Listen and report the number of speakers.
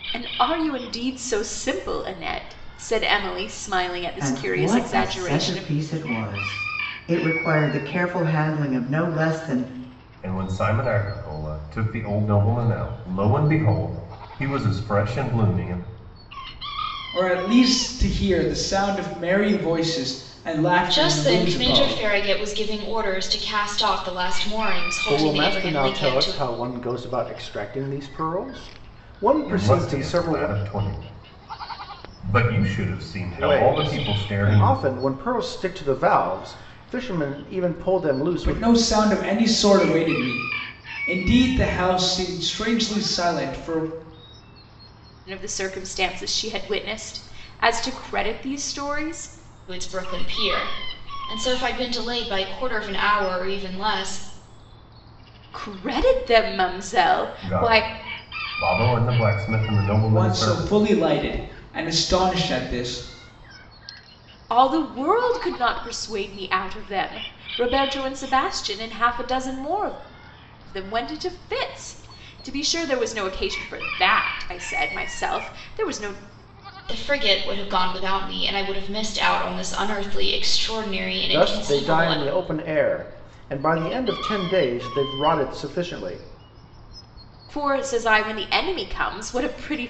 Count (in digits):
6